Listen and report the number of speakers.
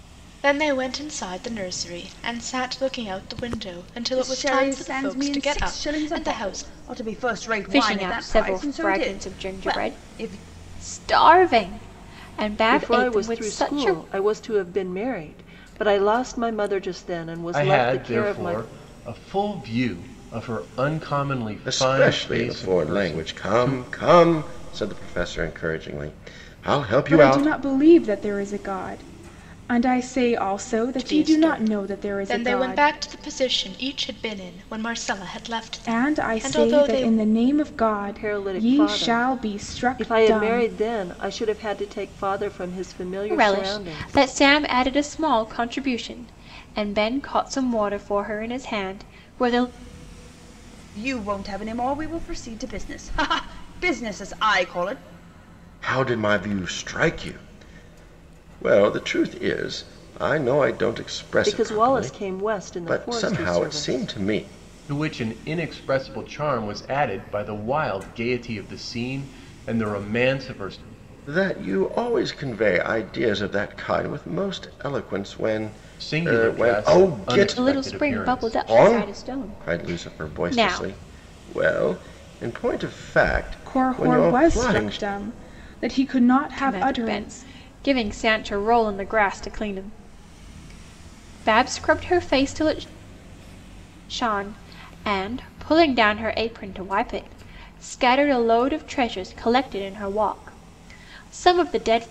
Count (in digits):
7